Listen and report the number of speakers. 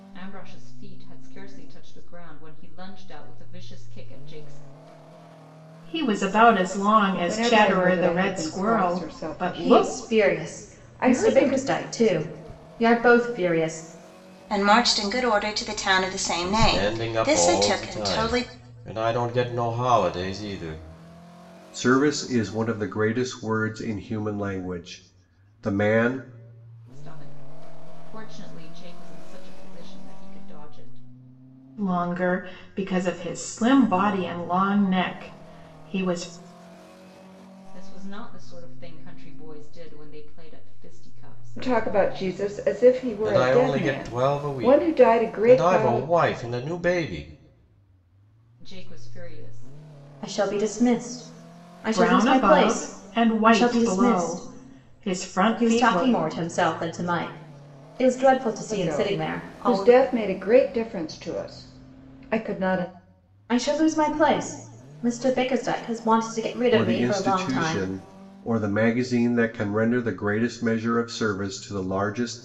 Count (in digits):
7